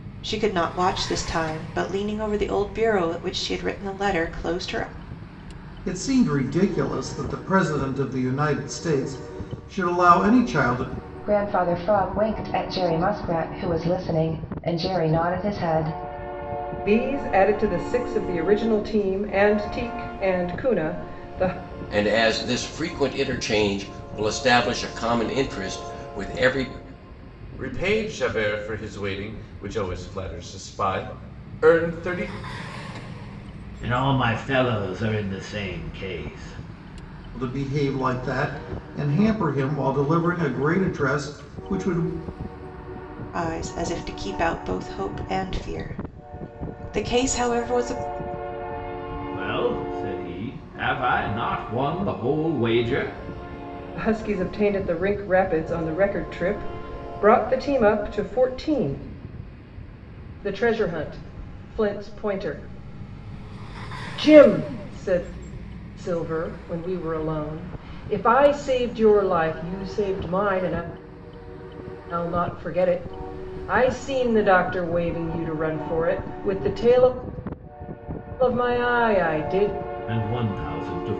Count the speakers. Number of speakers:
seven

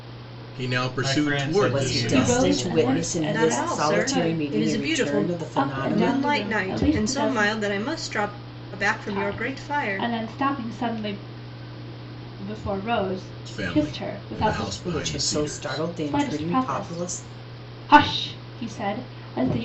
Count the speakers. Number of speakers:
five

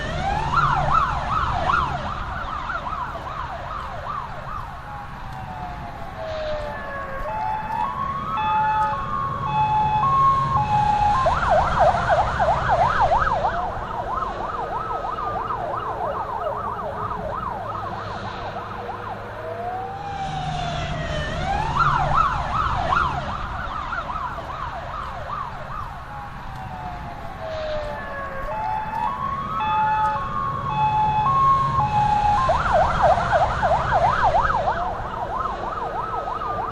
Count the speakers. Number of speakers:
zero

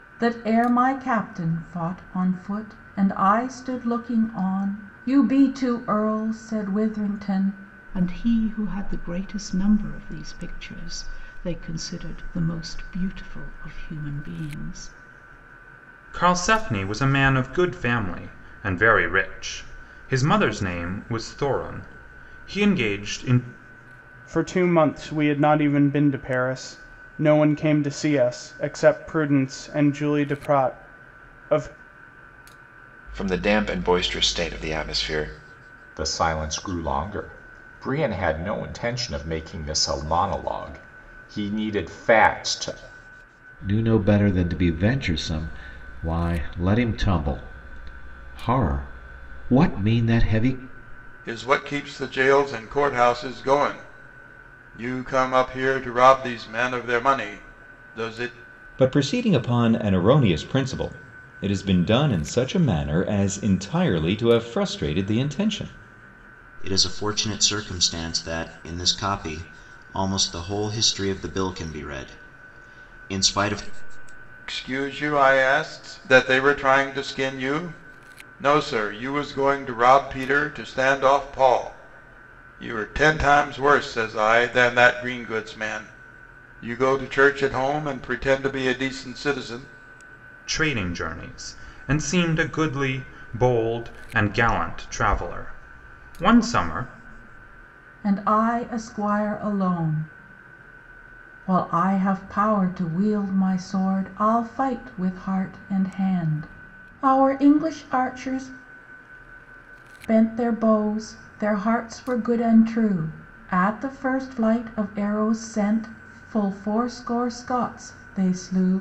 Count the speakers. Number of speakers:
ten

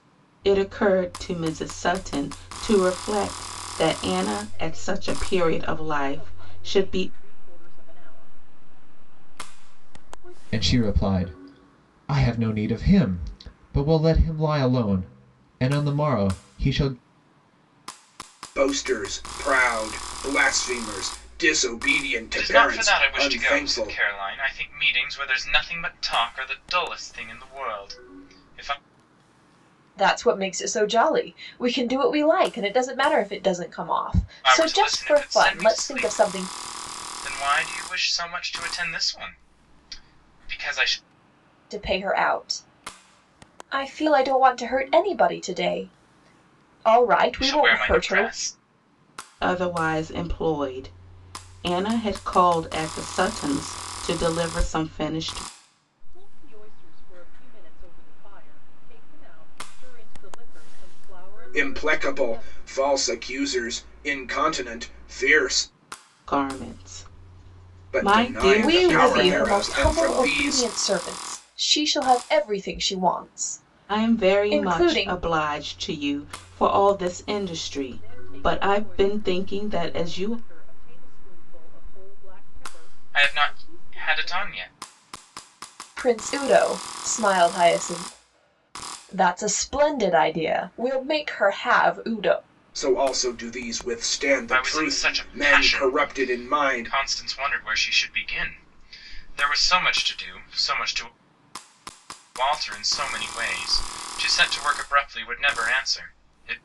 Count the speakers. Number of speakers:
six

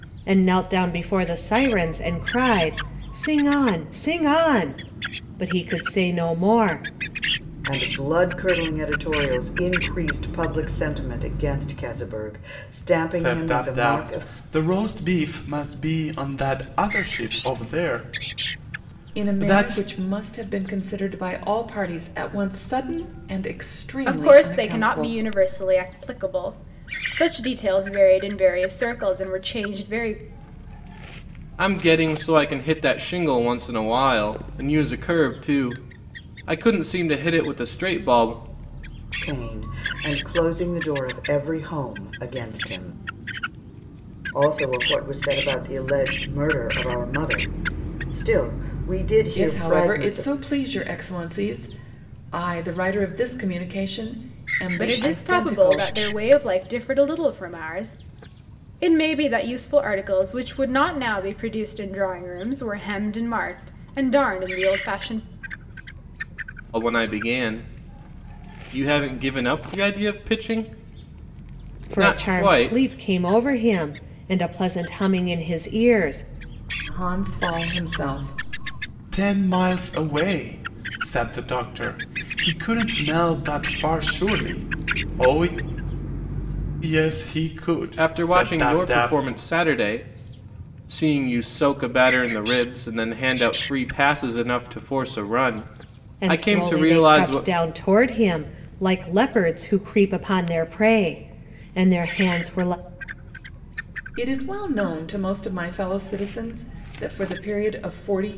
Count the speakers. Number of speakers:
six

